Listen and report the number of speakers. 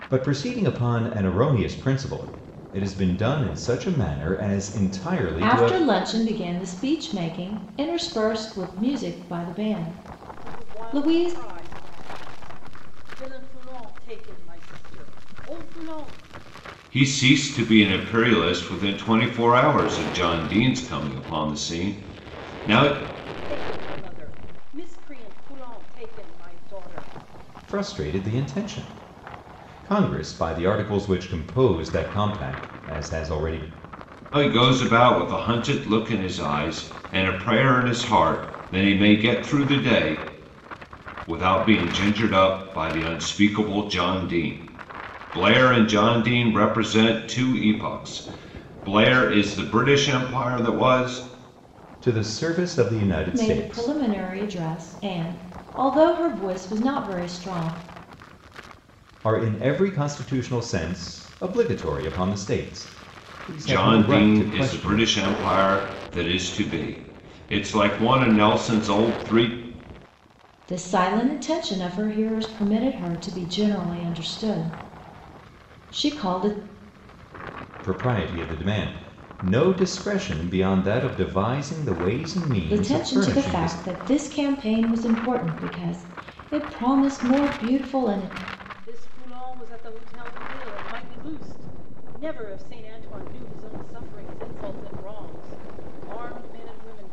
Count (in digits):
4